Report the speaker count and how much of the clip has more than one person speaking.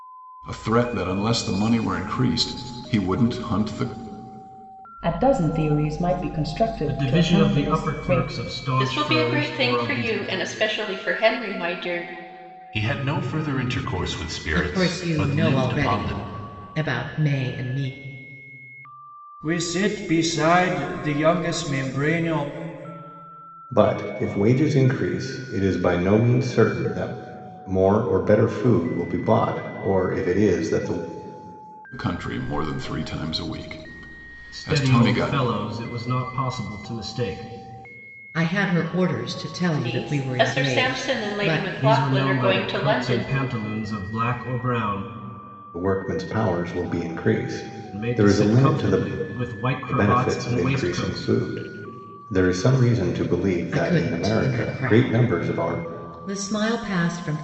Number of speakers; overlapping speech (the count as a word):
eight, about 24%